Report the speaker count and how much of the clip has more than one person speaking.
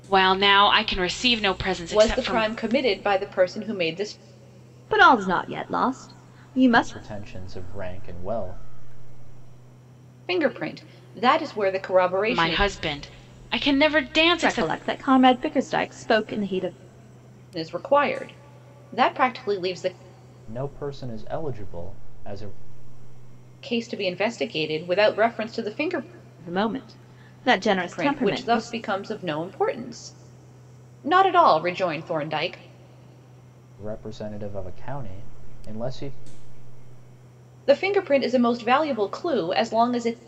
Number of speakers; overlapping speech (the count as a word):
four, about 6%